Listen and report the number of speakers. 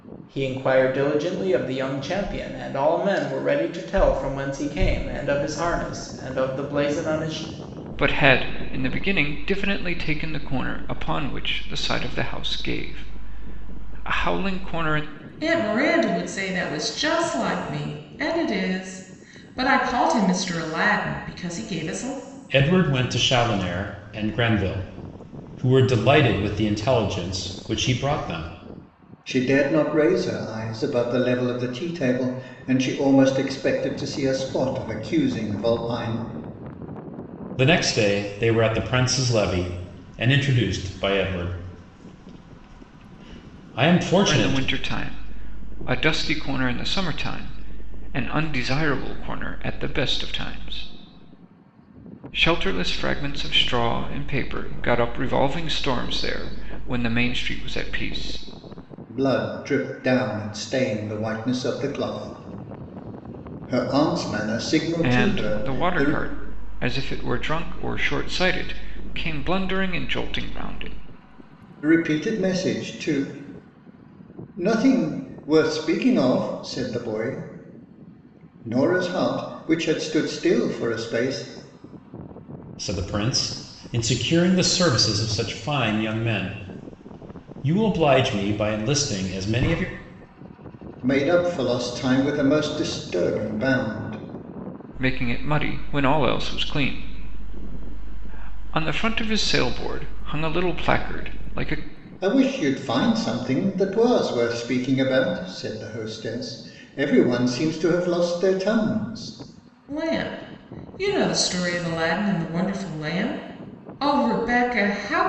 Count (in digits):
5